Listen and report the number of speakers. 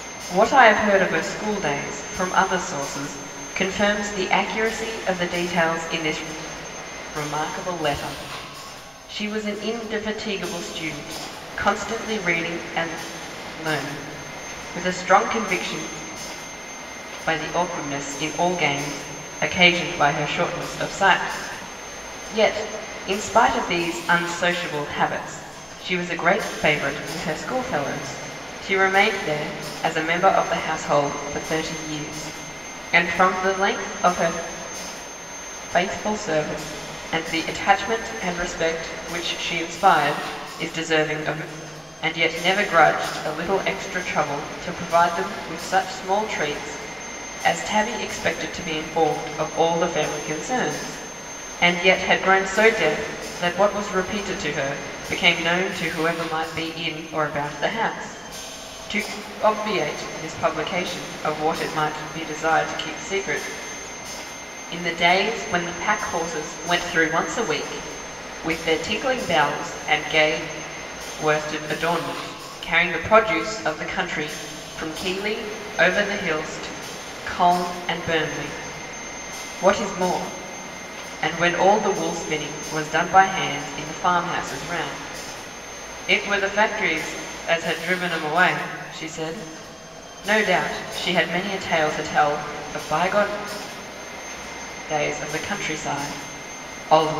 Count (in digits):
1